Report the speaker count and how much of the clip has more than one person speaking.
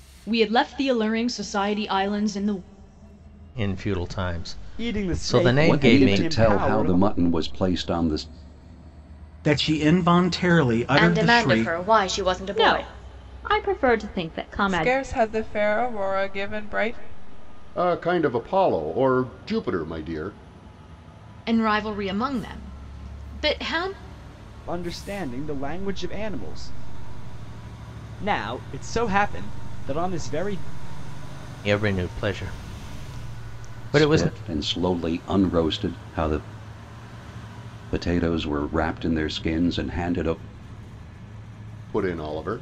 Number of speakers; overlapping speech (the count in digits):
10, about 10%